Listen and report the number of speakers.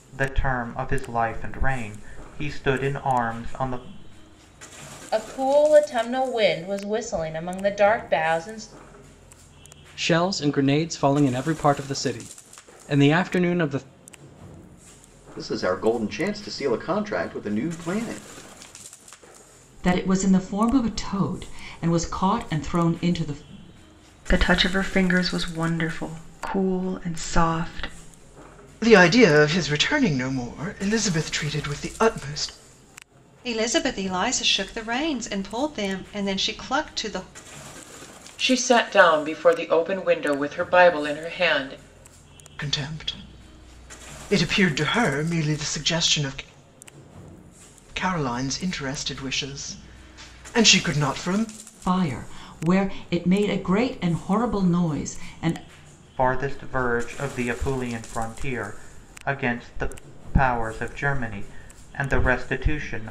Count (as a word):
nine